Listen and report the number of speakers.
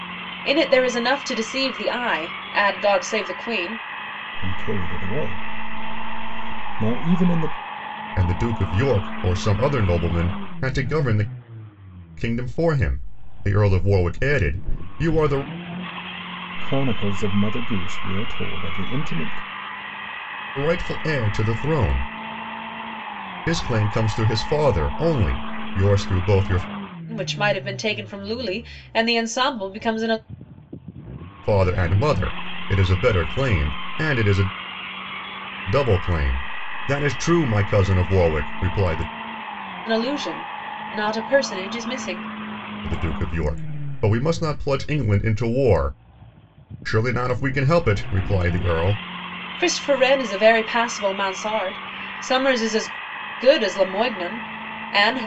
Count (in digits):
3